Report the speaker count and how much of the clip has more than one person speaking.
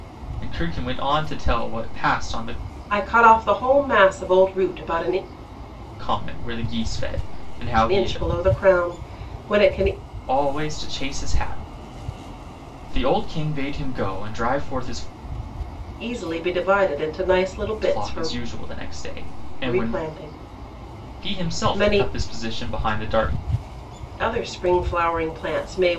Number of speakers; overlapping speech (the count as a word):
two, about 8%